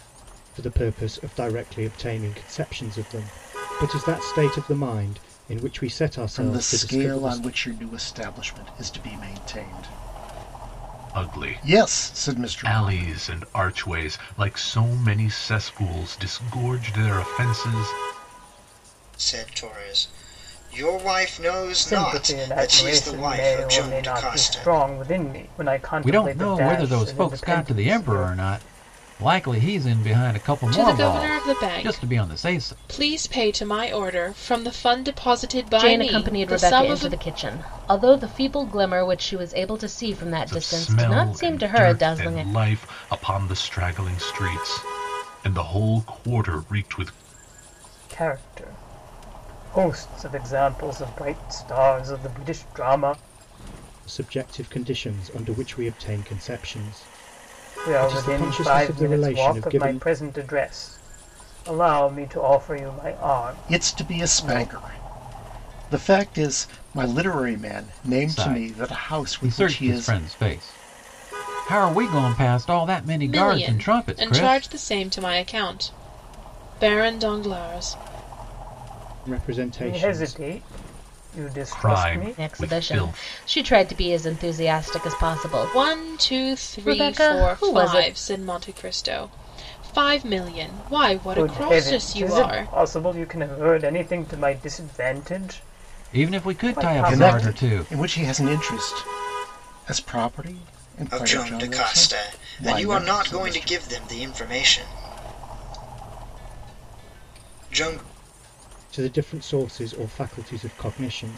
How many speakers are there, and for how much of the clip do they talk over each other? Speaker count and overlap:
8, about 28%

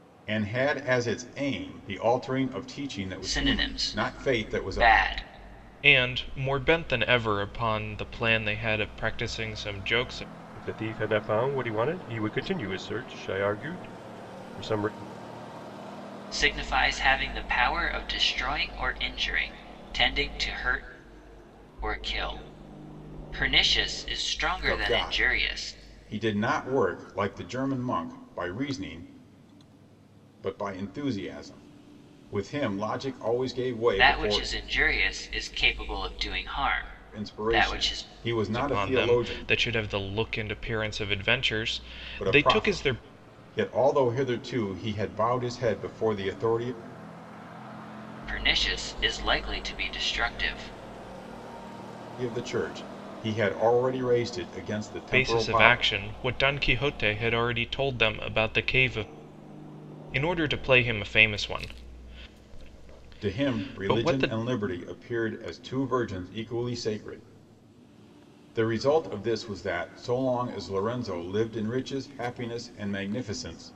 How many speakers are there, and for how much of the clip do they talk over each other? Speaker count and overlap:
4, about 11%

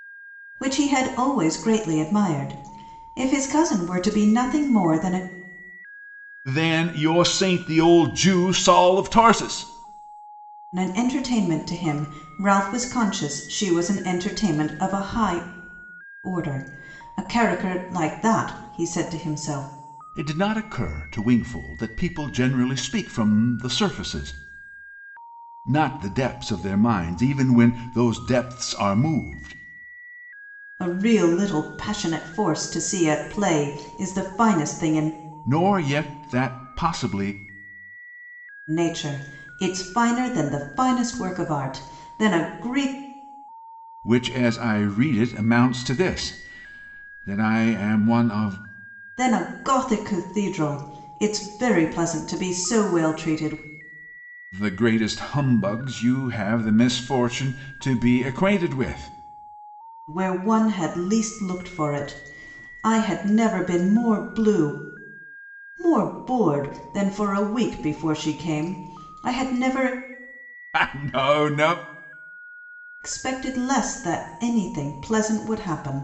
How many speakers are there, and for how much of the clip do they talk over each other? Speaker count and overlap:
2, no overlap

